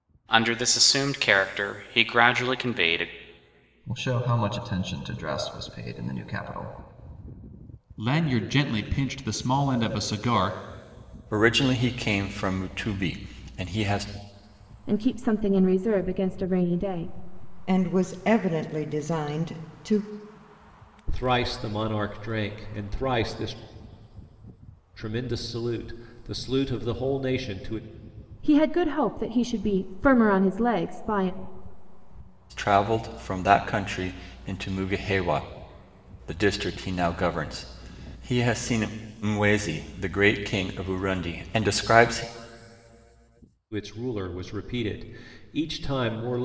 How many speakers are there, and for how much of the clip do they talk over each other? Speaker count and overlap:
seven, no overlap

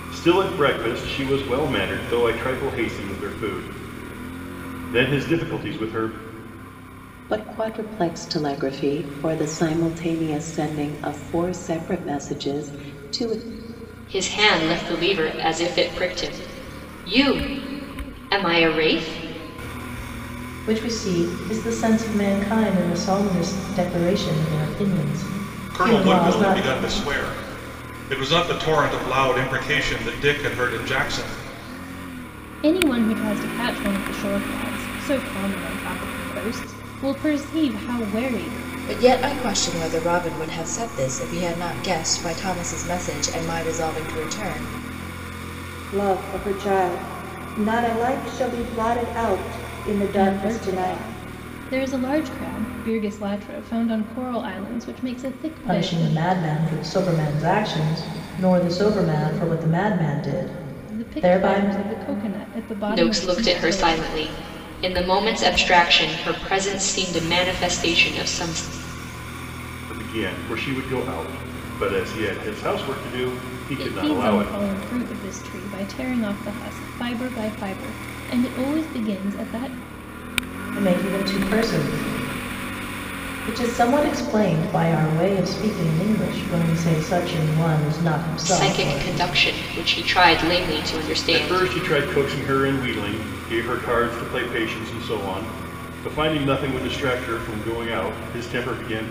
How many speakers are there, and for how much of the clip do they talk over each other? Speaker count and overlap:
eight, about 7%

